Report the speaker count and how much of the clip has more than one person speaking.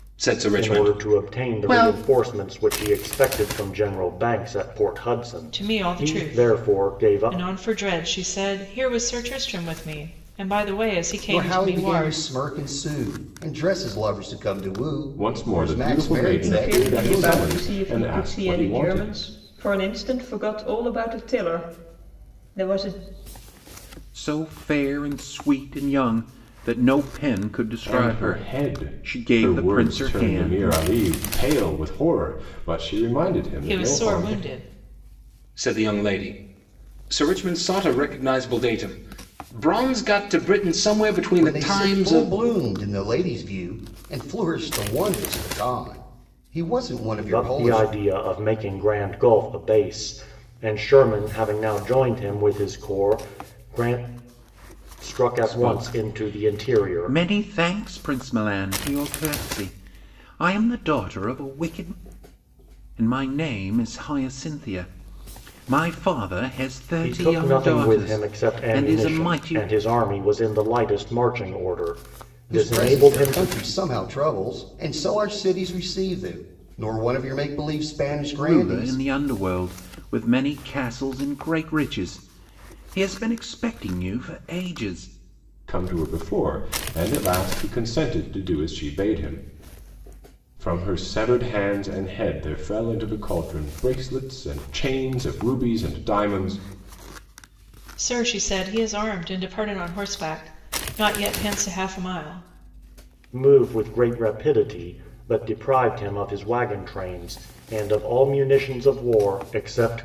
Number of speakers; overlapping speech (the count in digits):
7, about 18%